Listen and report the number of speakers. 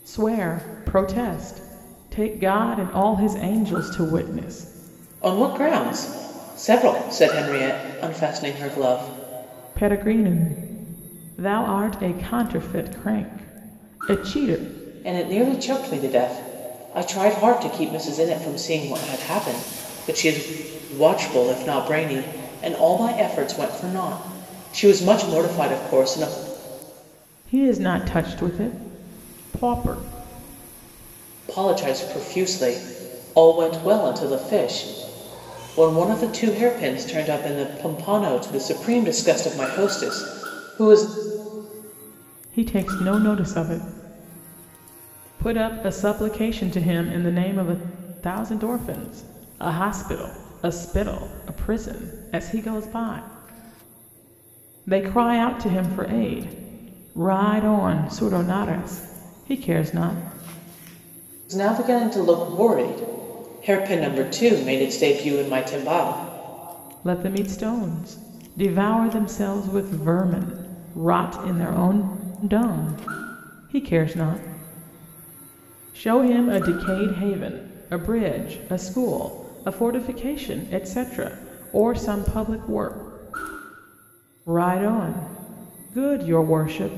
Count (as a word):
two